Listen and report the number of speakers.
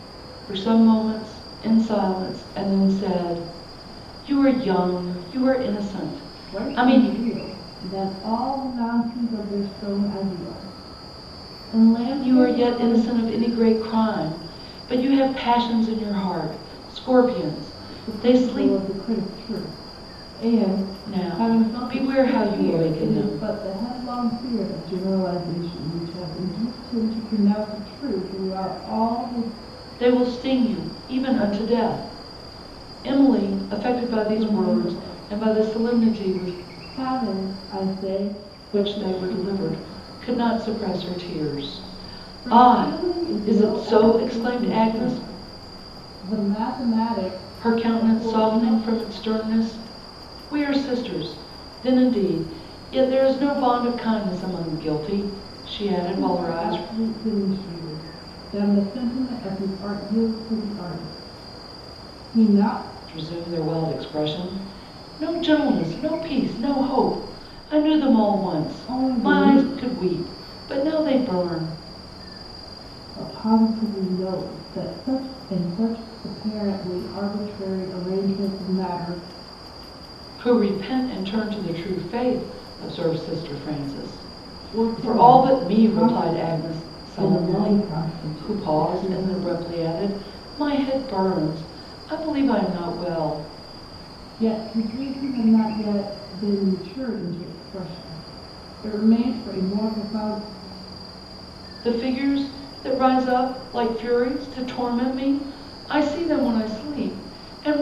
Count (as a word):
two